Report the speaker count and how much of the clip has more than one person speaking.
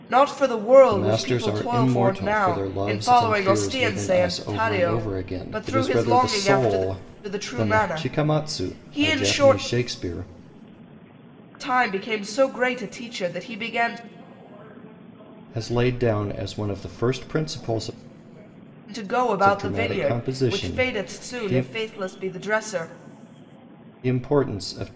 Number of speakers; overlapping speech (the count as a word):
two, about 43%